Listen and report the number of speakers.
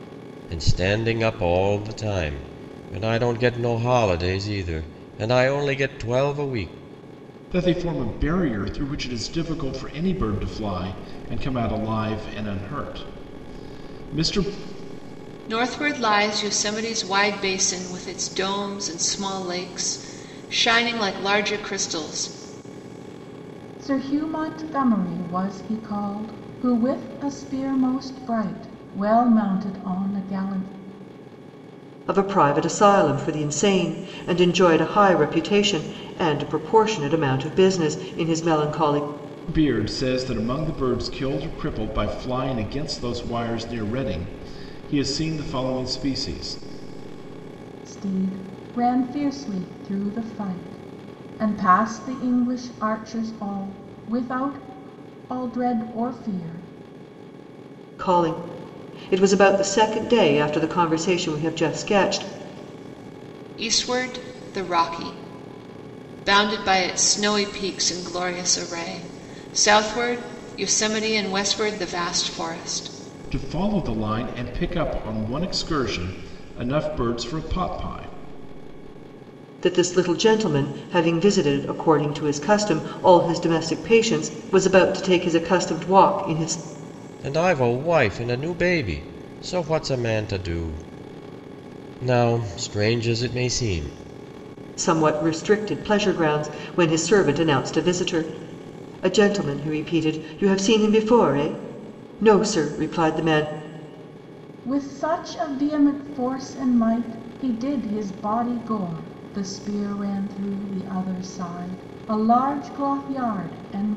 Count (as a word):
five